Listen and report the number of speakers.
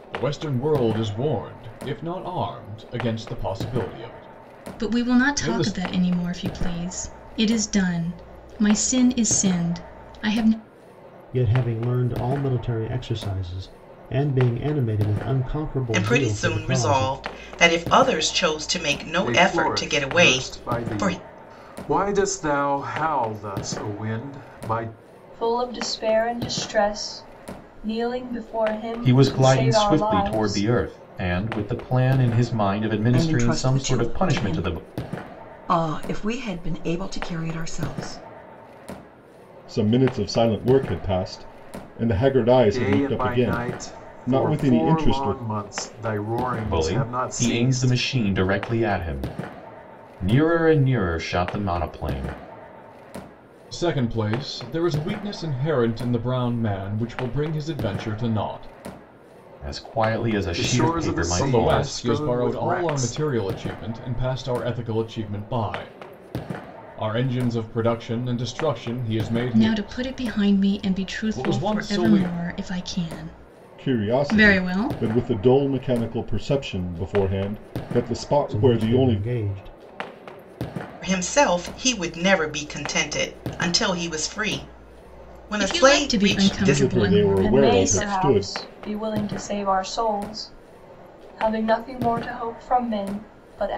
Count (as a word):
nine